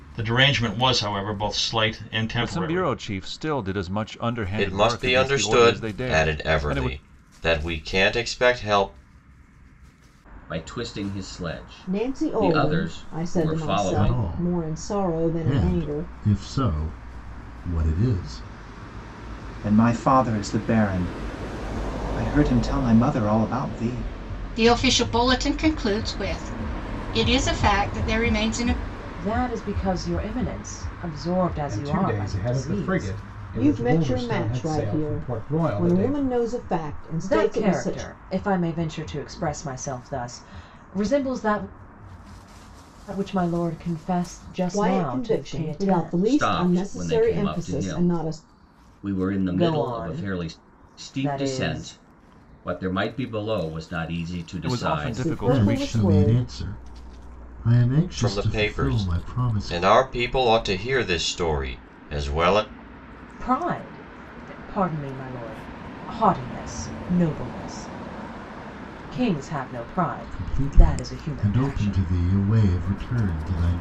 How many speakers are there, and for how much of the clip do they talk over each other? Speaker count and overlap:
10, about 32%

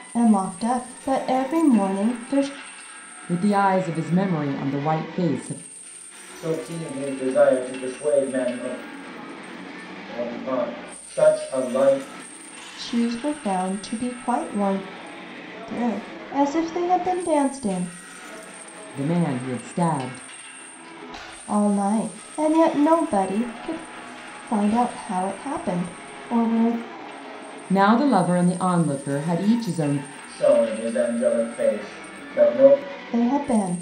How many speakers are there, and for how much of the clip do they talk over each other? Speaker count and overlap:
3, no overlap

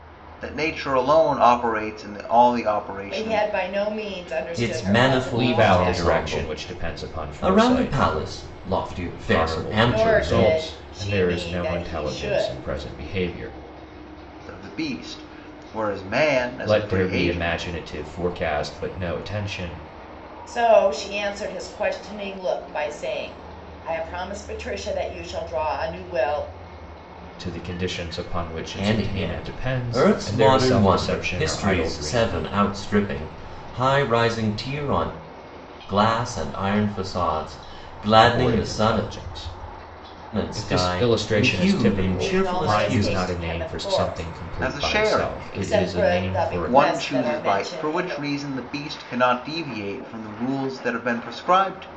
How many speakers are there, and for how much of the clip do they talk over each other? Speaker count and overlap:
4, about 38%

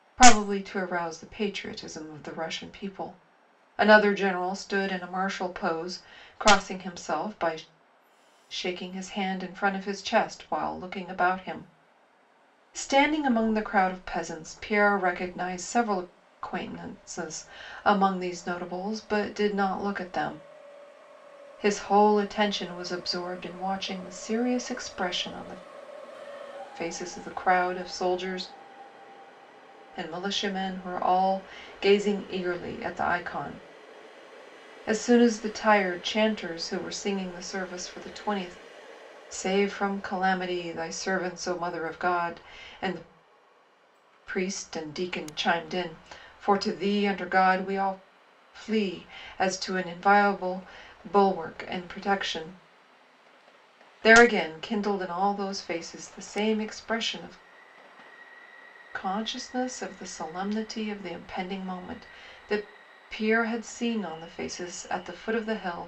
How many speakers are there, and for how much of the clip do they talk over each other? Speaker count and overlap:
1, no overlap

